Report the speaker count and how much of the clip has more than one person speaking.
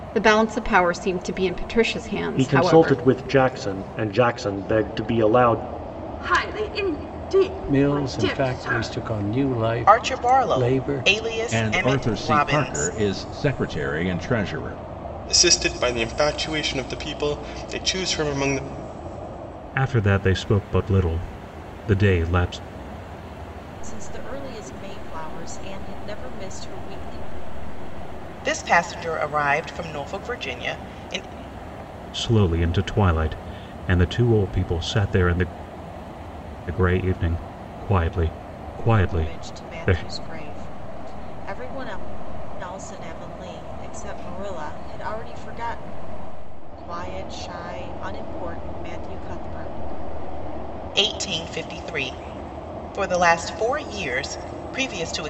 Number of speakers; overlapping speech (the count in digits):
9, about 11%